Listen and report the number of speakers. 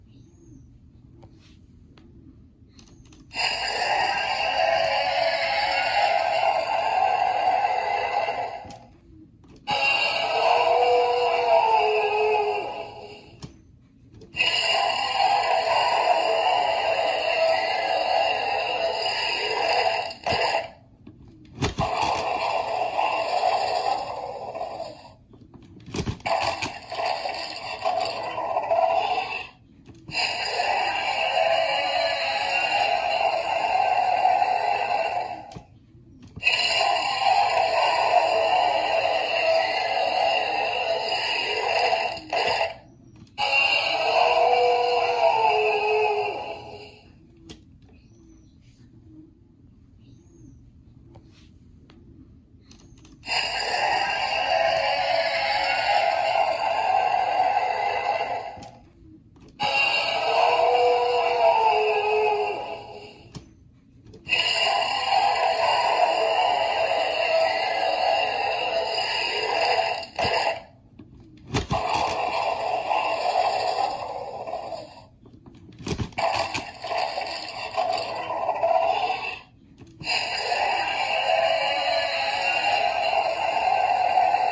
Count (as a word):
zero